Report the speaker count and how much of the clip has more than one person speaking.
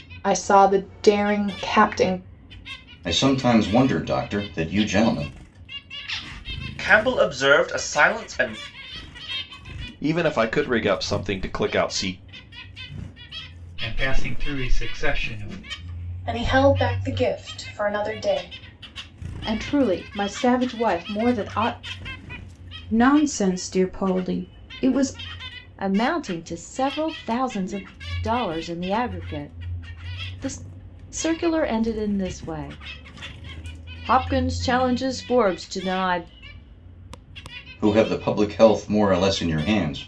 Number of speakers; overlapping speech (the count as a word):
nine, no overlap